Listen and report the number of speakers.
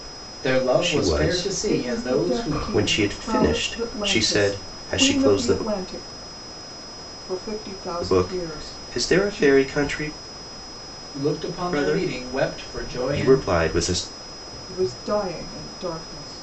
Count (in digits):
3